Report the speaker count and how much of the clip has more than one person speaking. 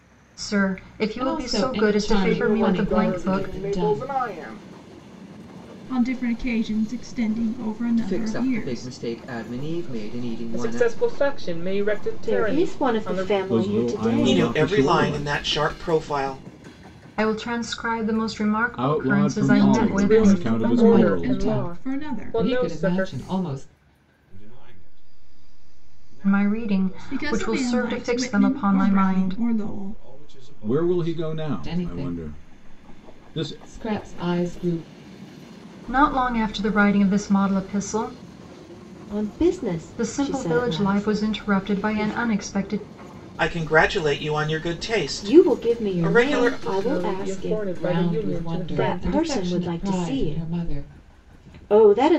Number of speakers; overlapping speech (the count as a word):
ten, about 56%